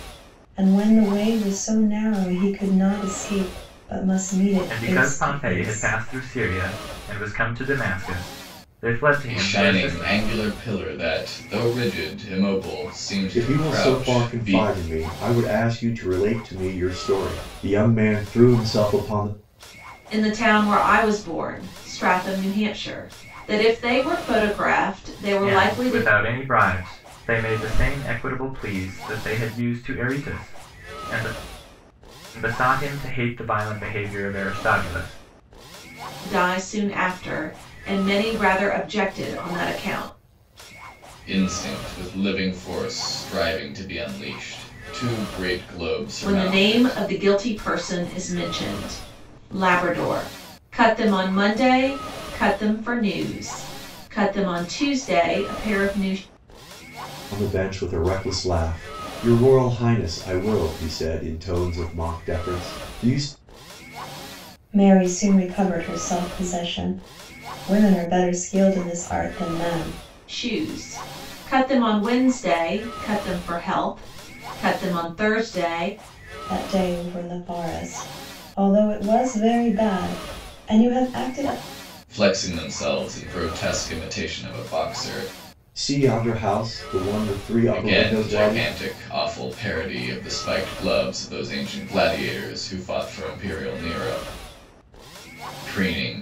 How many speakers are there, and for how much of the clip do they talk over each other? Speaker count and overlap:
five, about 7%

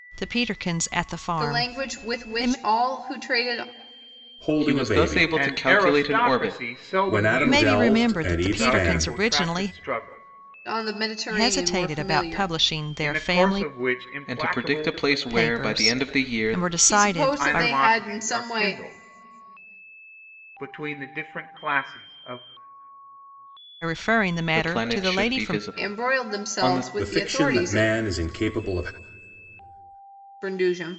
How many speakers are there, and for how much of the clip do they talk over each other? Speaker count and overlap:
five, about 50%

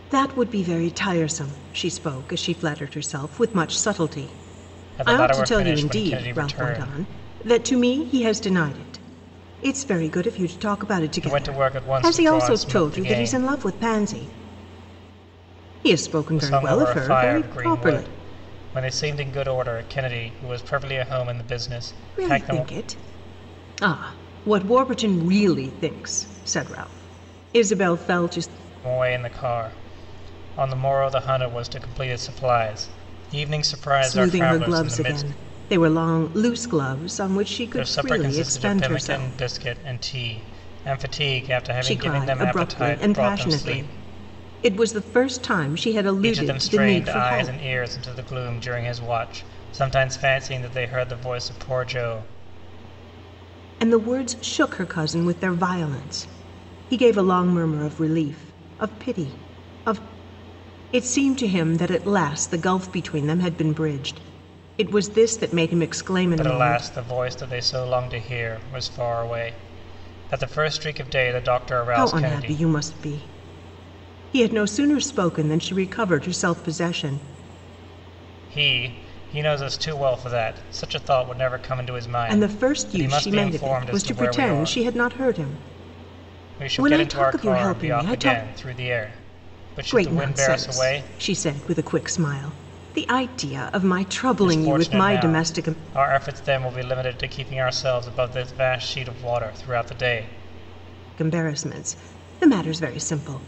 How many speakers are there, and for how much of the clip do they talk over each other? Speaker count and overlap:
two, about 21%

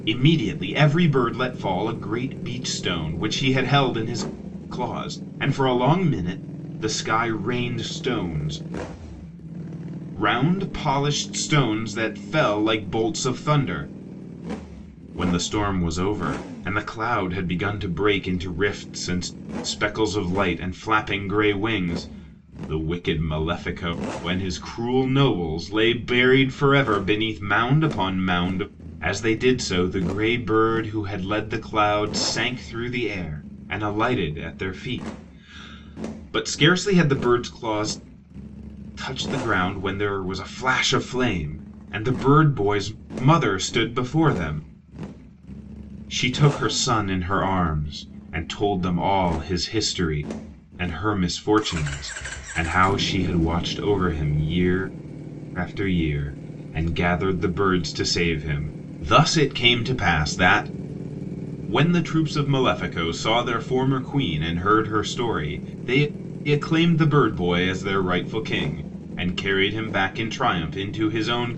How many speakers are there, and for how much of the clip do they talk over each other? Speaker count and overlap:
one, no overlap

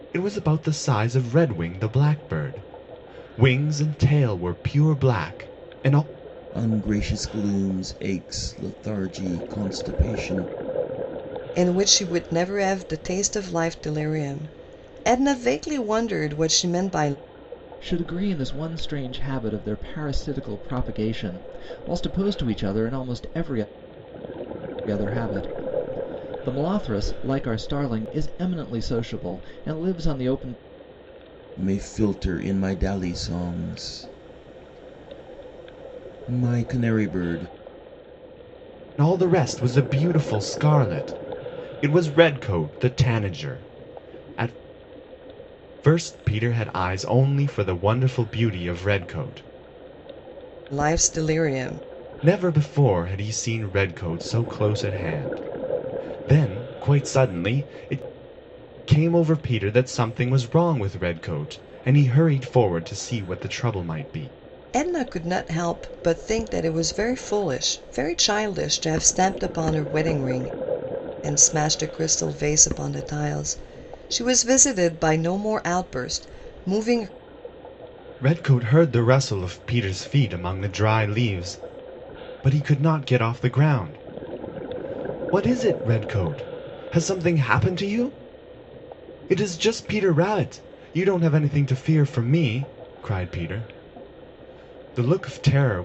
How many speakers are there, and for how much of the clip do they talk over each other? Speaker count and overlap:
four, no overlap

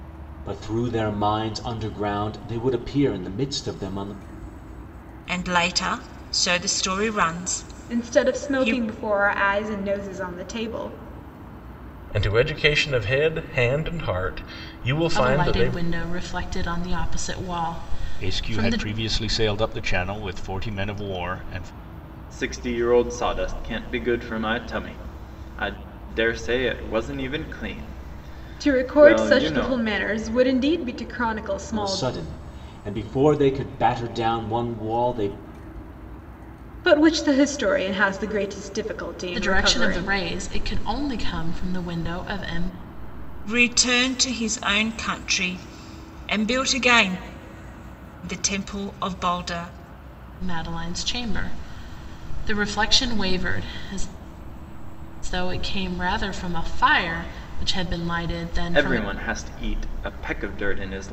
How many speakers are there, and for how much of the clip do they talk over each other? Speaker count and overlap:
seven, about 8%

